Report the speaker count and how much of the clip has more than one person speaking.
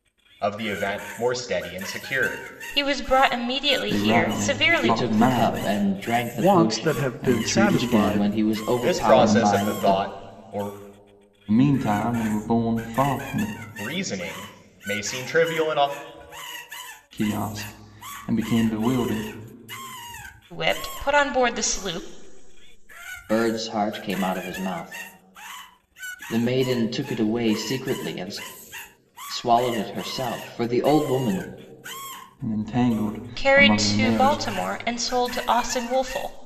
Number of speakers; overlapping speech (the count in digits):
5, about 18%